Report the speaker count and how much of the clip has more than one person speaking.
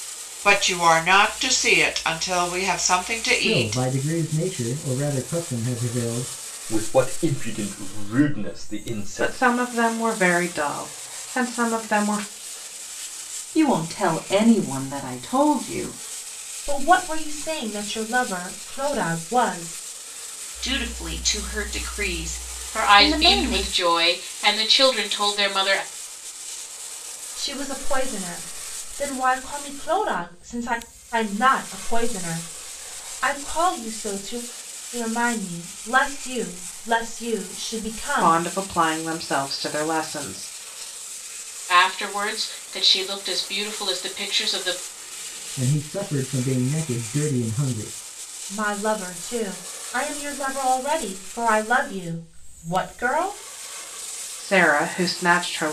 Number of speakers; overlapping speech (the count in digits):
8, about 4%